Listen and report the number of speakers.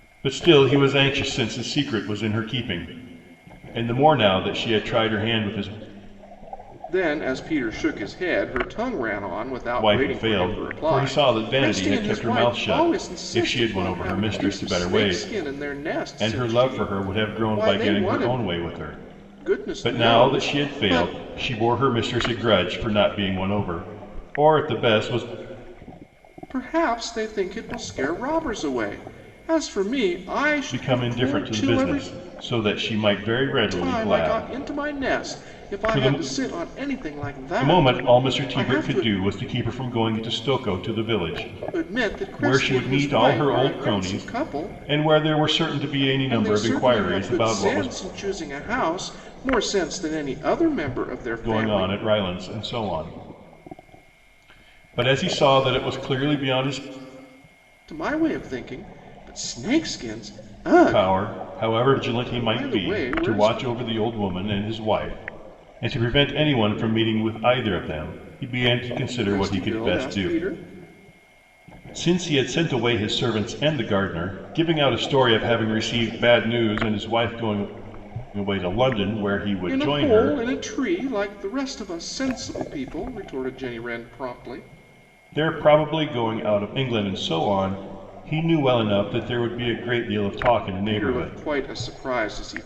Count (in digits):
2